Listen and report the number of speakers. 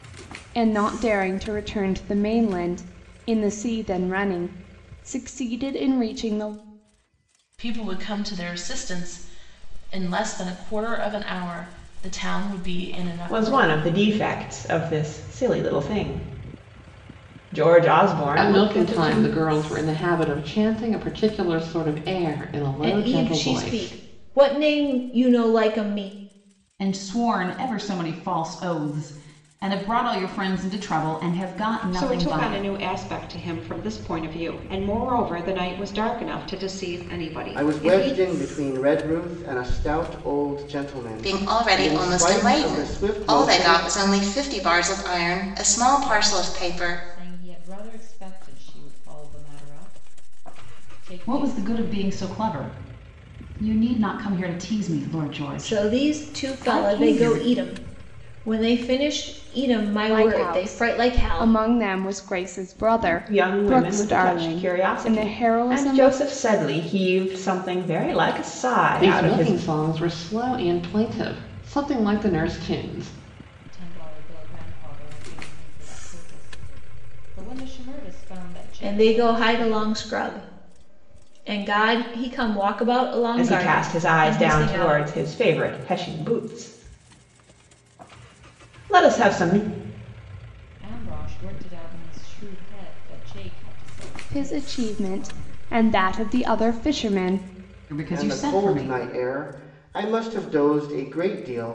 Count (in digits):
10